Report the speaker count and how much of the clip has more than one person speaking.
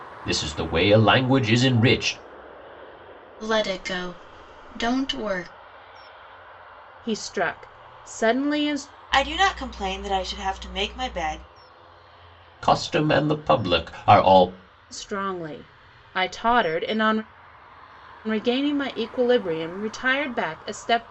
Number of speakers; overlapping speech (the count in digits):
4, no overlap